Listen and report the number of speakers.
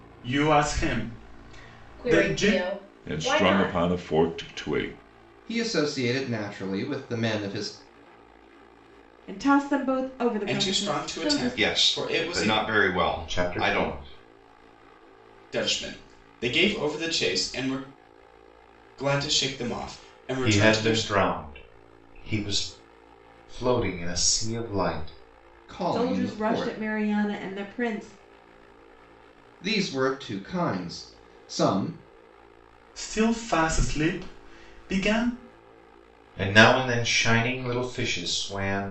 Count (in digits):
8